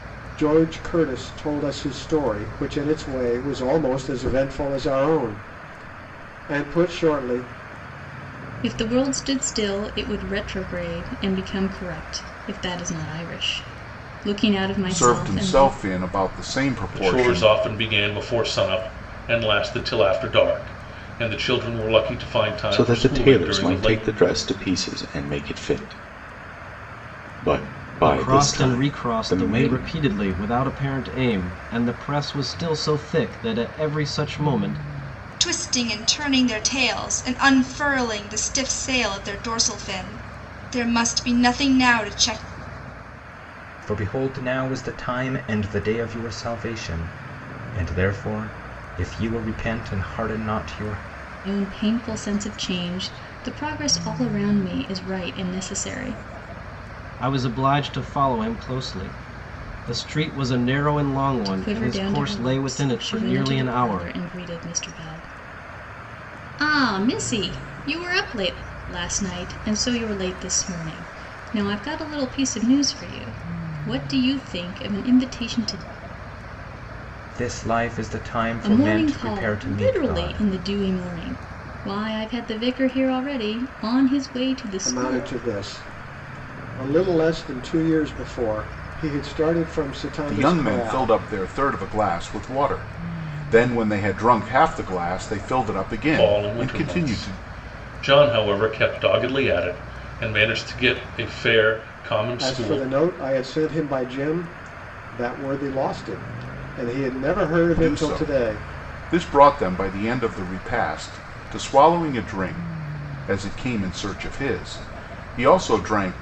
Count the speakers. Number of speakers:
8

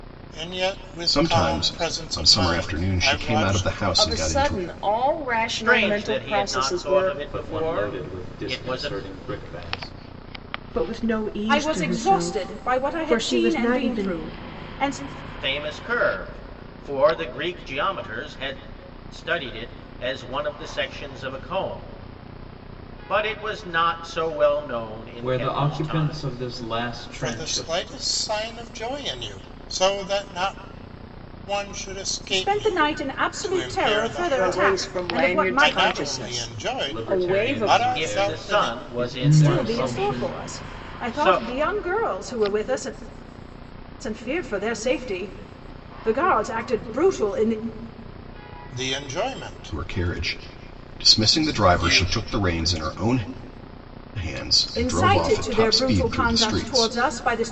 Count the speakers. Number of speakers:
7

